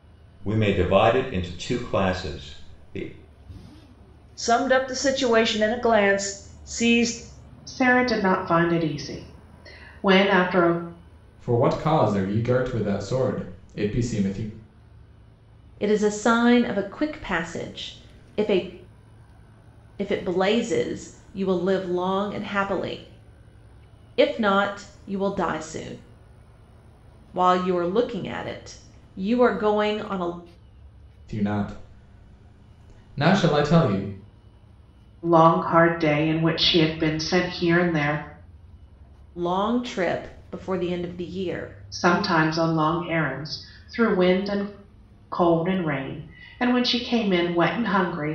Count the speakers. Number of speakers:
five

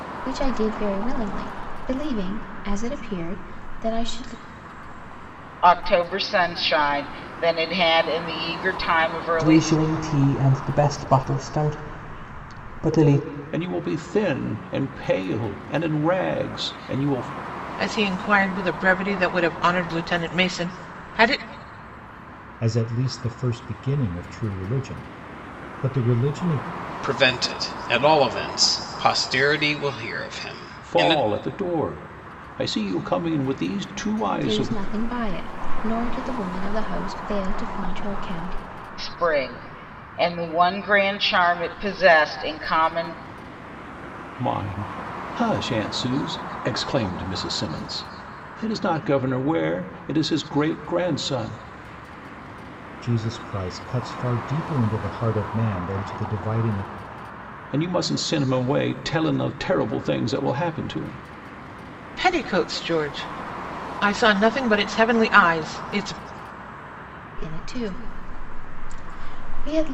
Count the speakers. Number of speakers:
seven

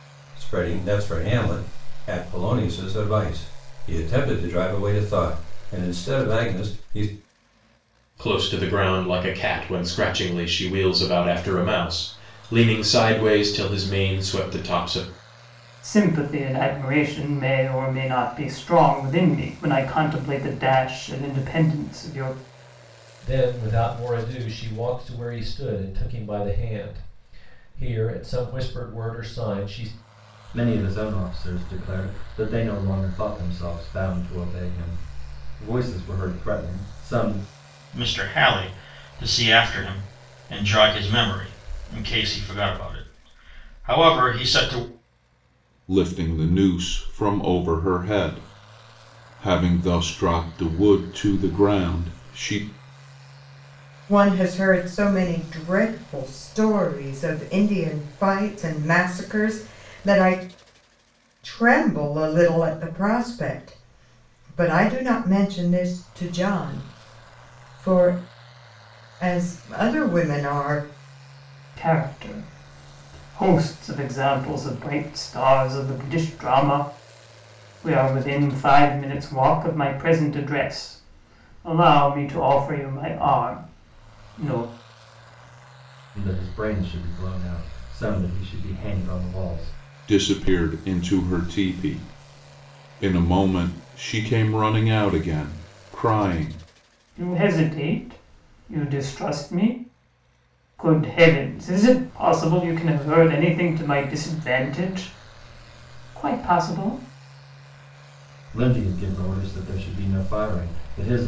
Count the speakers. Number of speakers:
eight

